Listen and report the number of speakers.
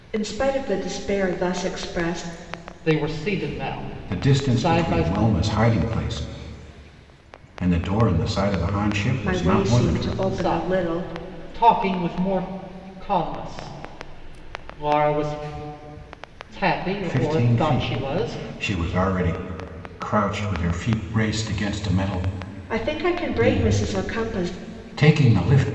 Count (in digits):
3